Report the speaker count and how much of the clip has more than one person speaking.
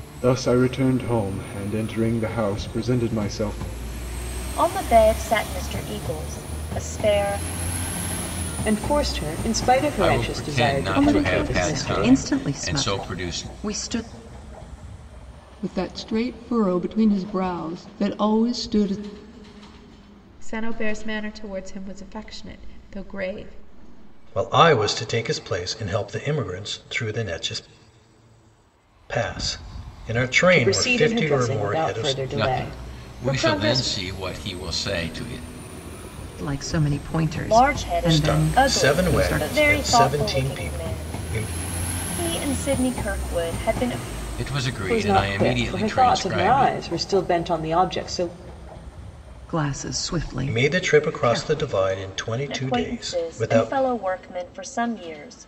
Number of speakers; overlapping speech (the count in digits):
8, about 28%